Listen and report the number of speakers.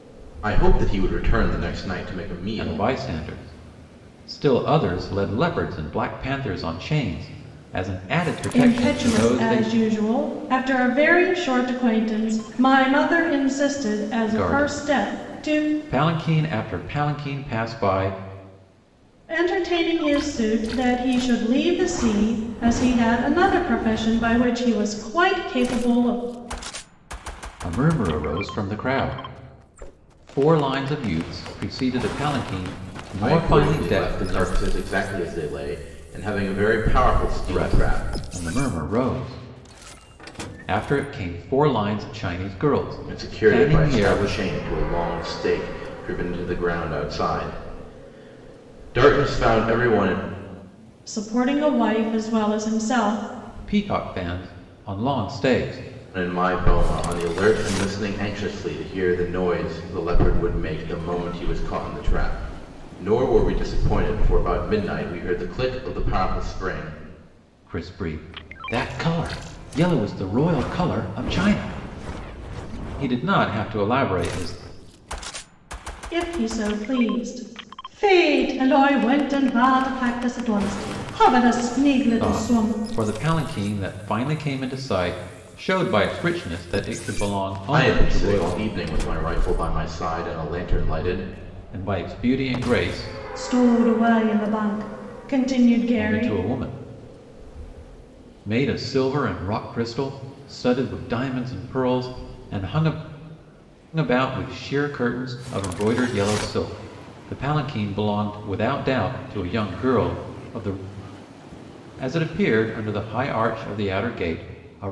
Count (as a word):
three